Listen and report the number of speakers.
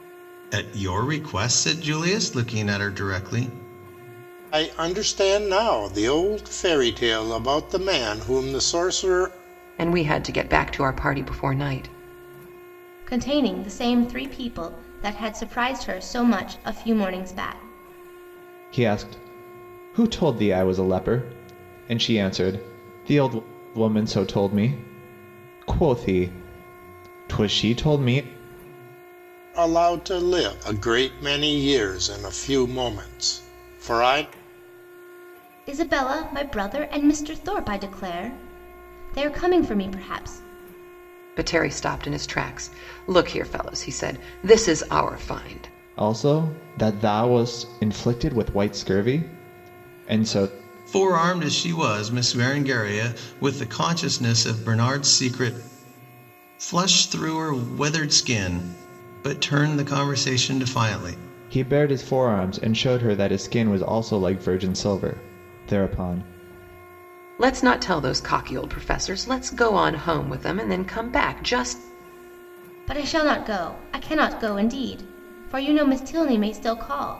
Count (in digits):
5